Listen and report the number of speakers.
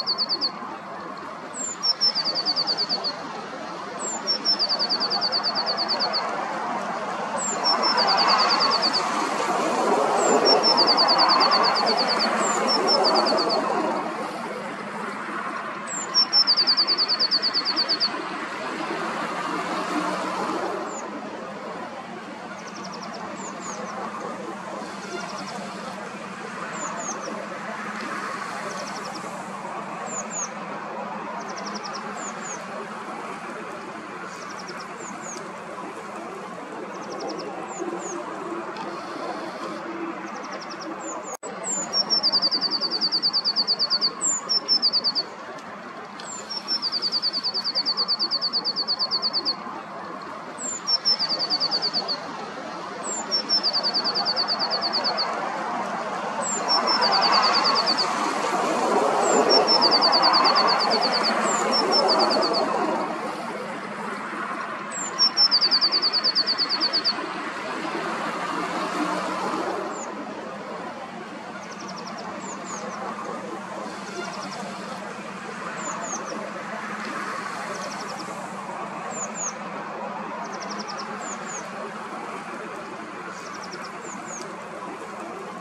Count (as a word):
zero